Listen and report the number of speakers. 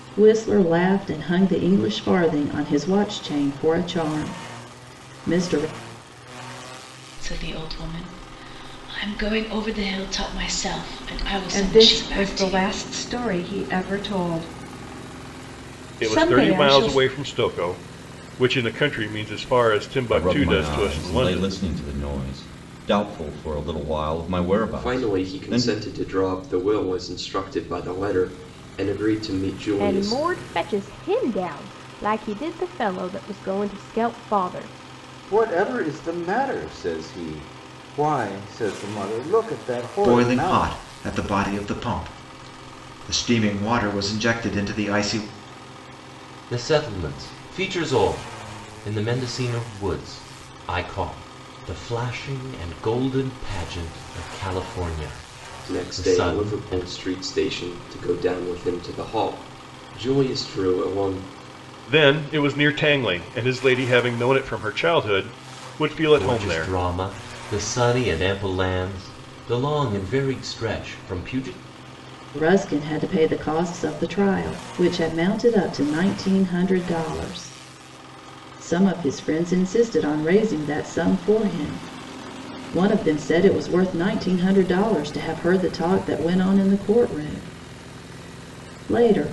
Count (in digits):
10